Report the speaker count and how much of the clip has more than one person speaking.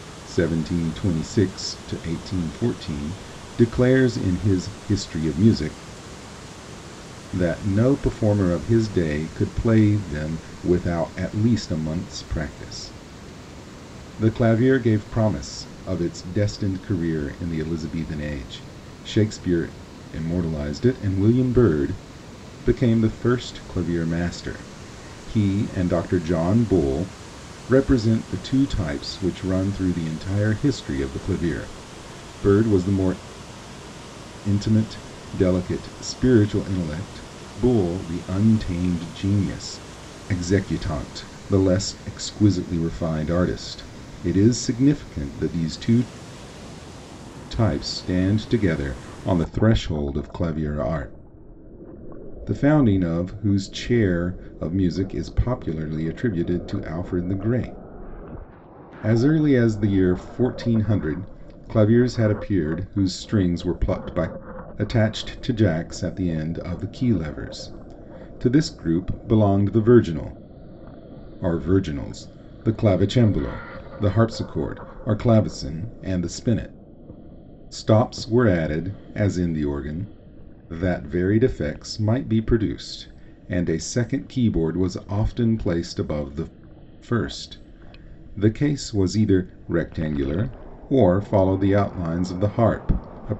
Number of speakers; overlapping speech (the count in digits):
1, no overlap